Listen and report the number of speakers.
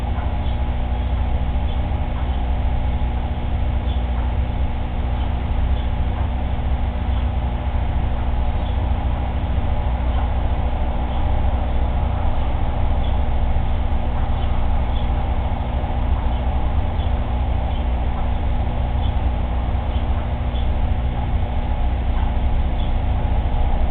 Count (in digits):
0